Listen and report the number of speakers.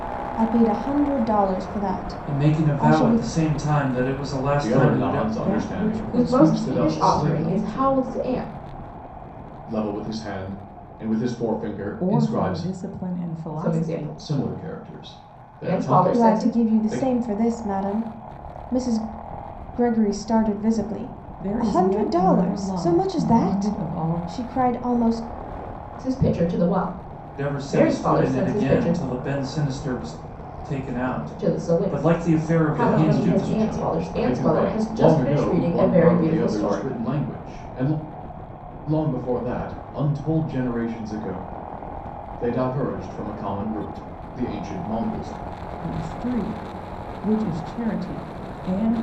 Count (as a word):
five